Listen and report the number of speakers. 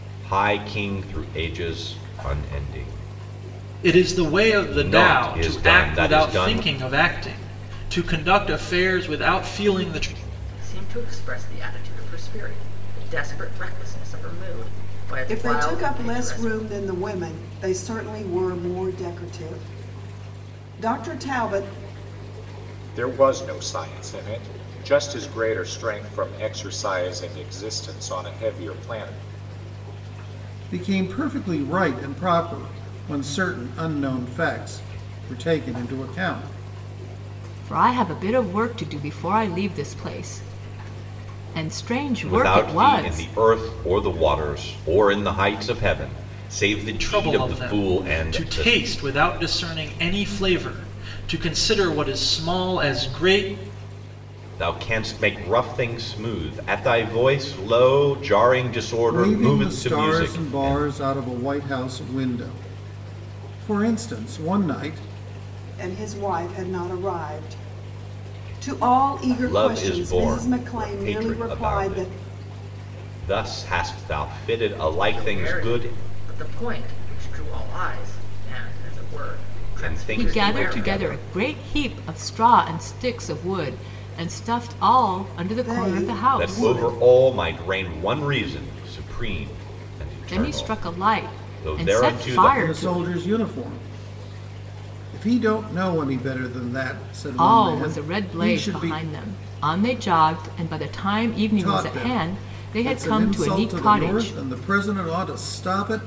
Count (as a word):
seven